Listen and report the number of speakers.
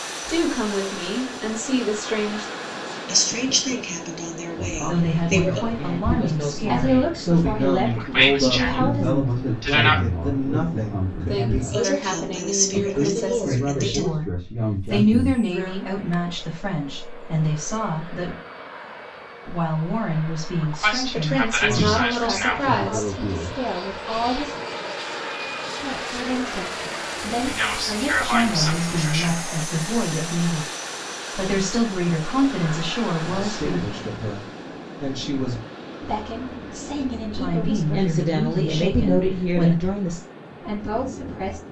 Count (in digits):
8